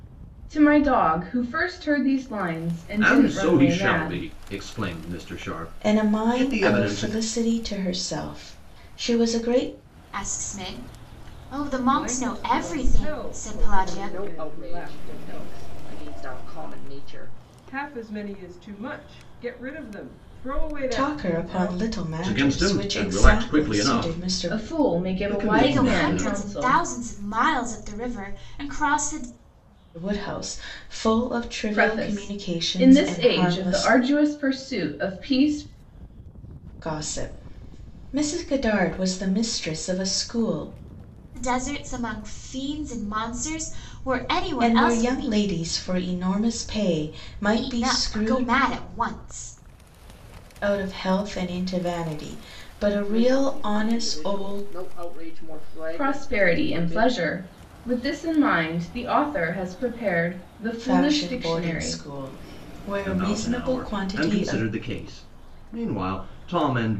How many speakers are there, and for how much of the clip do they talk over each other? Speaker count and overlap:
six, about 32%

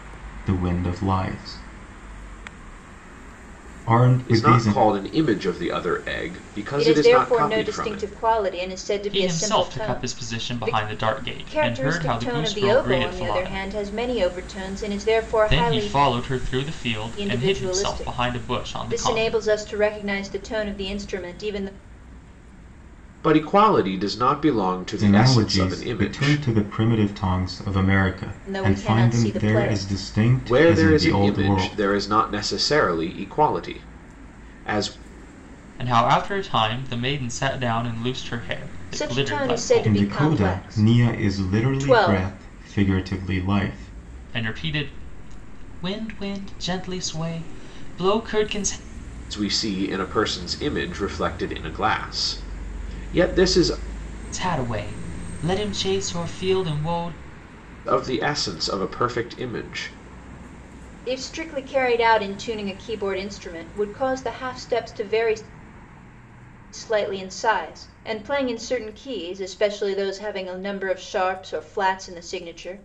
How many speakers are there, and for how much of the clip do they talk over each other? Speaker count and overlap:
four, about 23%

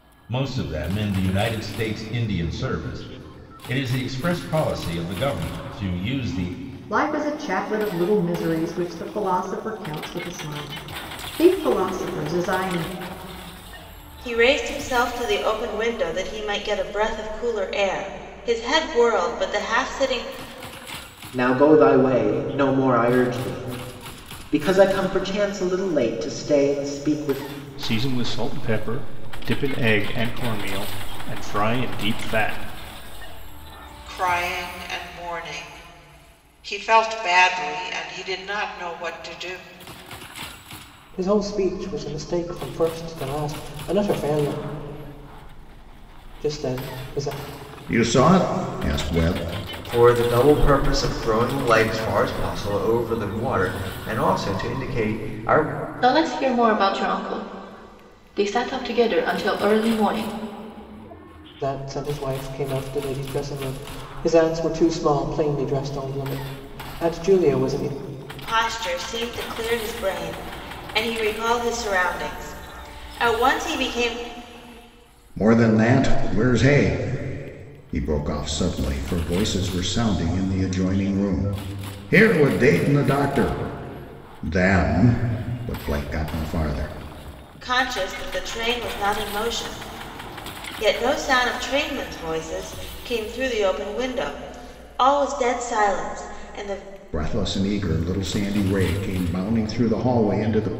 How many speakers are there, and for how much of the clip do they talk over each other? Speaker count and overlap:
ten, no overlap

